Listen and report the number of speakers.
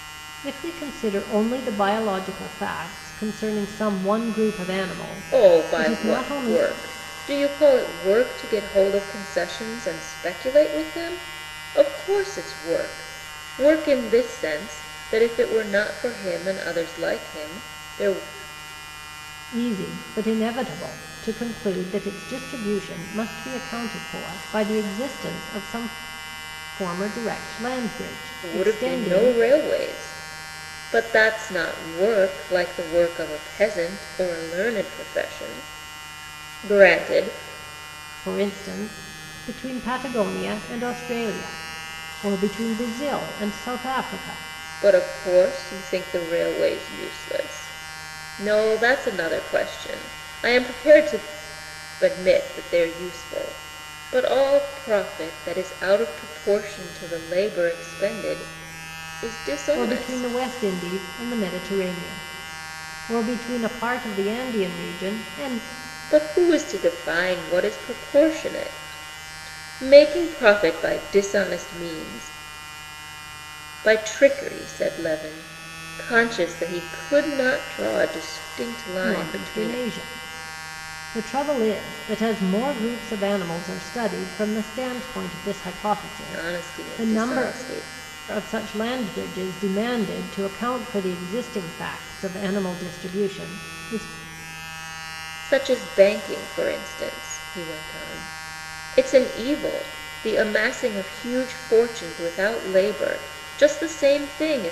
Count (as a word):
two